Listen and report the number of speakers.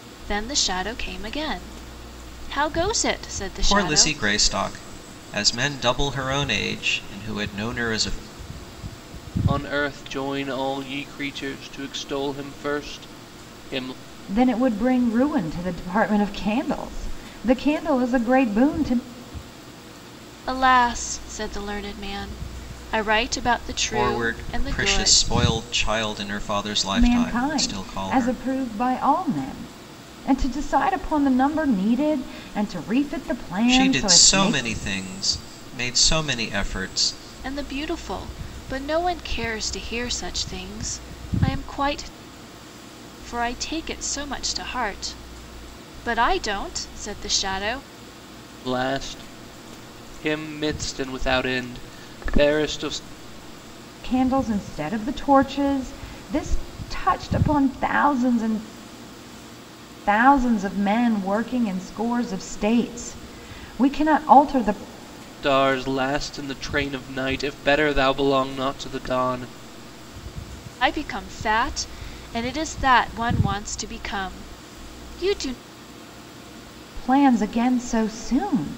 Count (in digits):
4